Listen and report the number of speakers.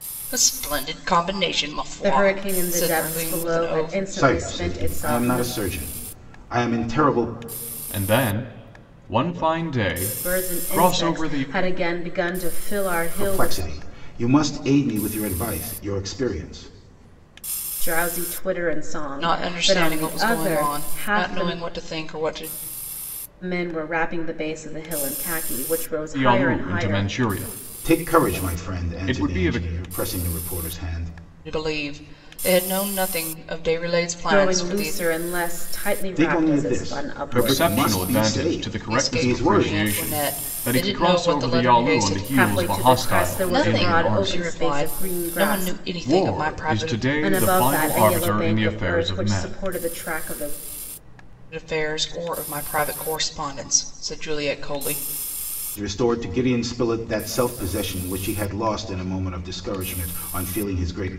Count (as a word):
four